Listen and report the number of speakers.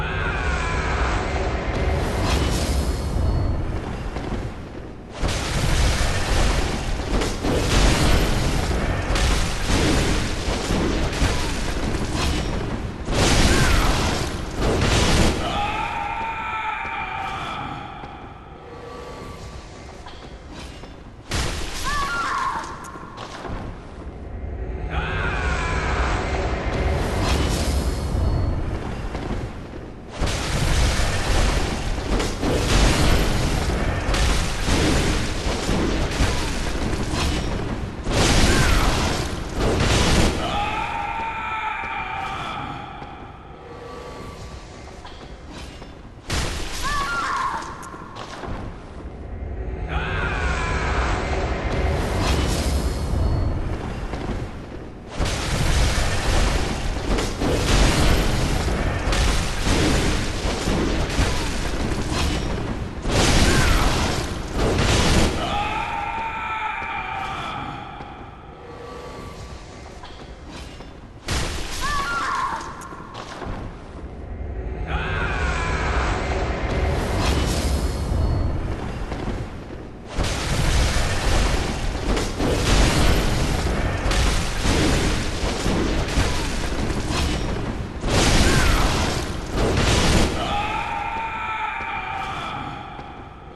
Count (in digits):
0